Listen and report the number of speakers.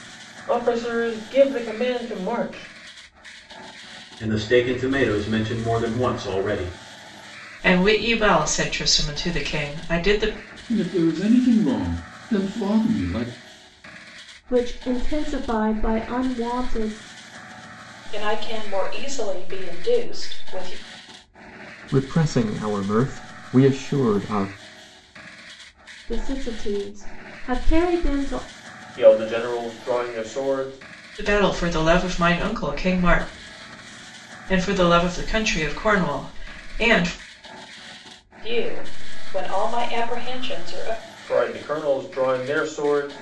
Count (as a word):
seven